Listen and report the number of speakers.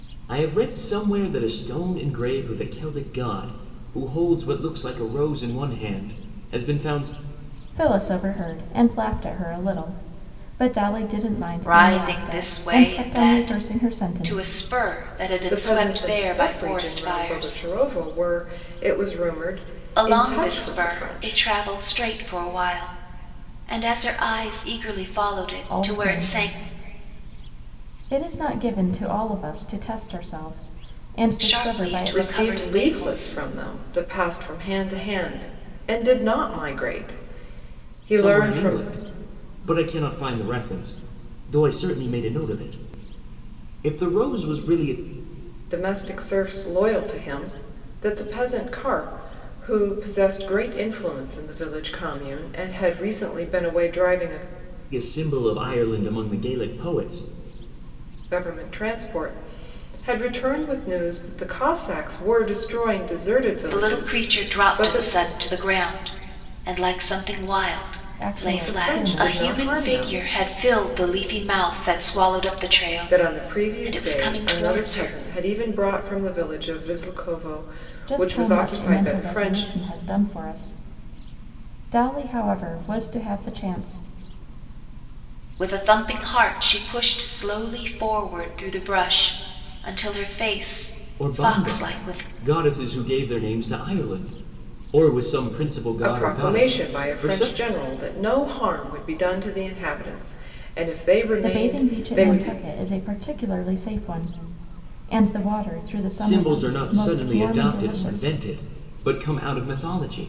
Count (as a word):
four